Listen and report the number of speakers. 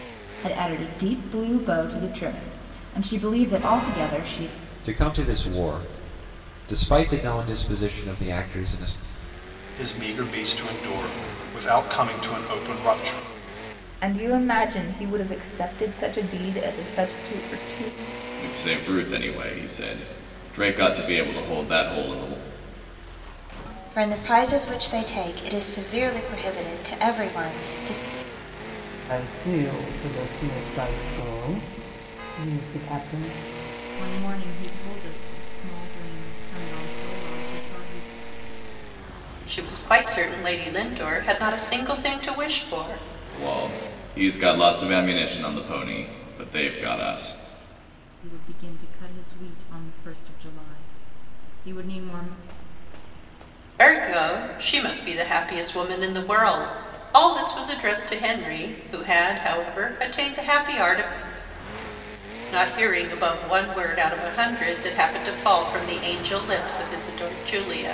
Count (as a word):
nine